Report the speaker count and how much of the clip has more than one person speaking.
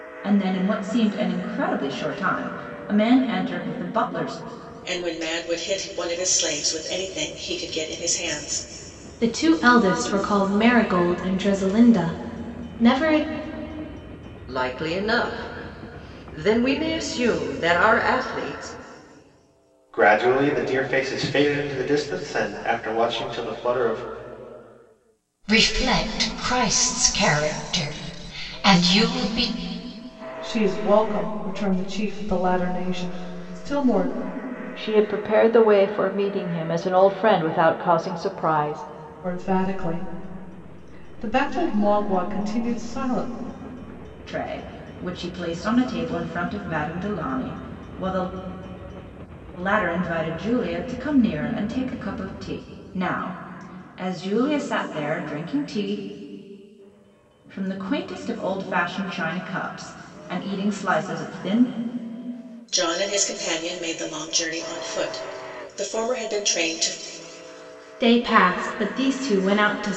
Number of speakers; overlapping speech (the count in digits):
8, no overlap